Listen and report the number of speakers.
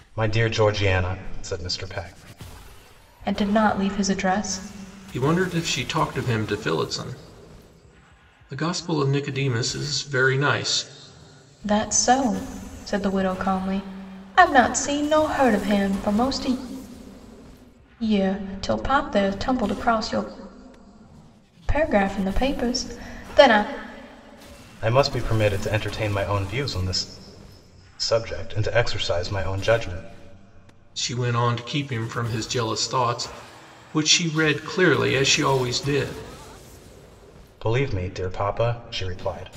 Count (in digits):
3